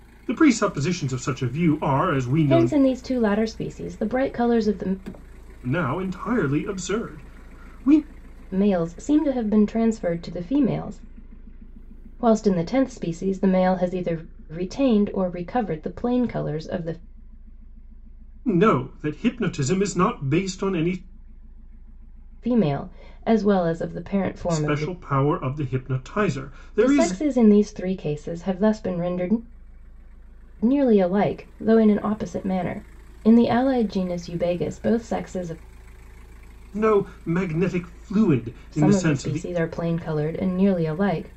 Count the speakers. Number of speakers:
two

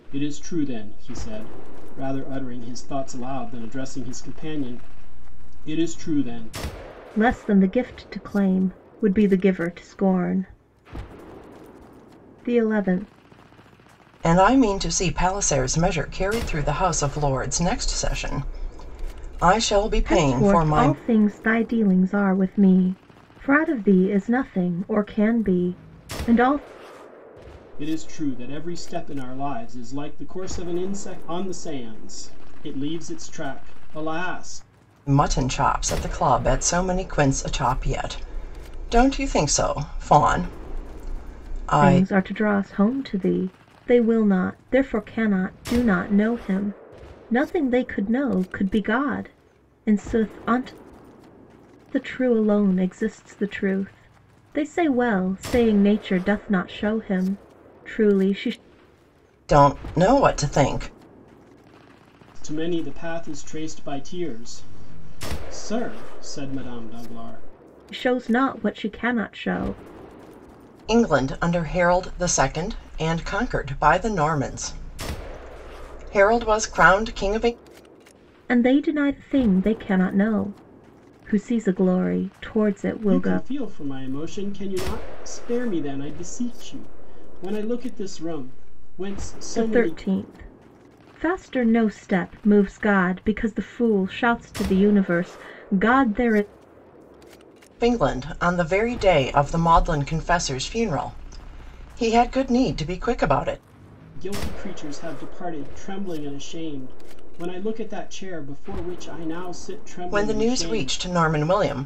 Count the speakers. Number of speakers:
three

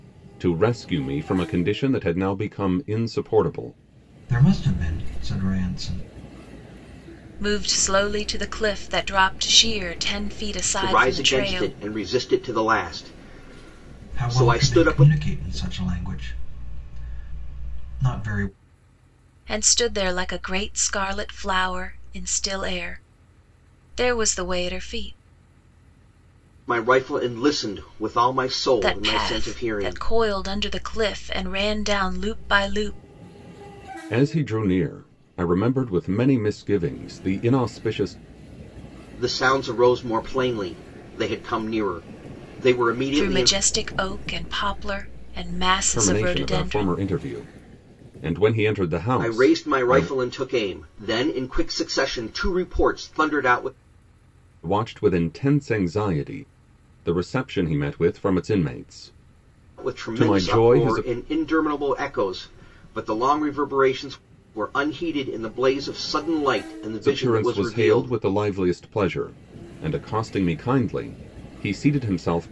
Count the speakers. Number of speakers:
four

